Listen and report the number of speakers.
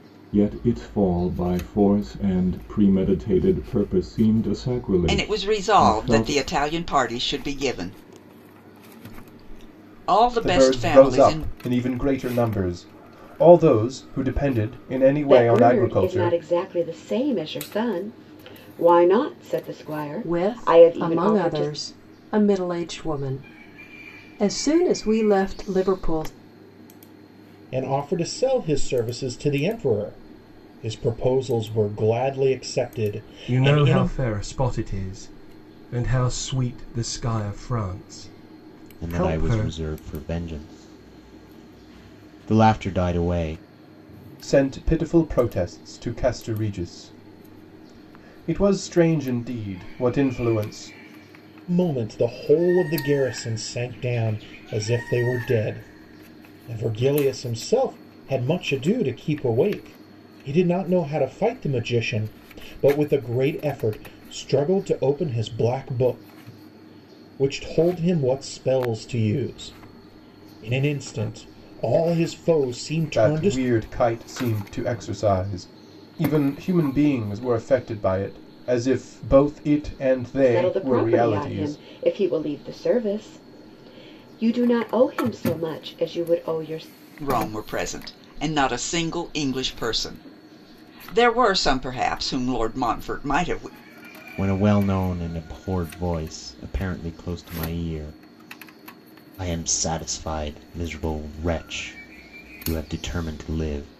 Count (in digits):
8